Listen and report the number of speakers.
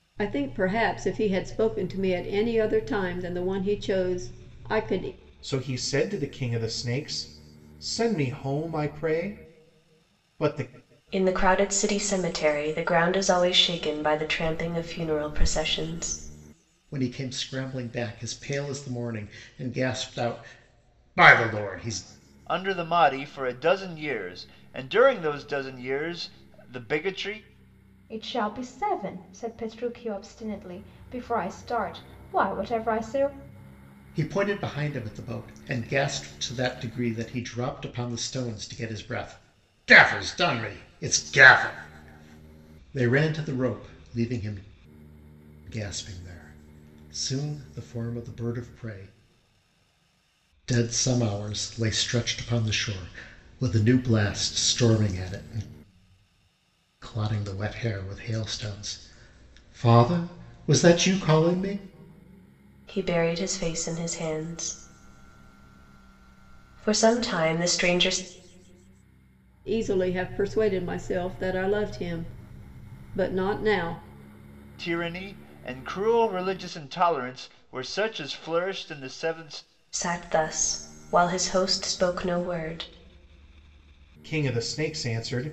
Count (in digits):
6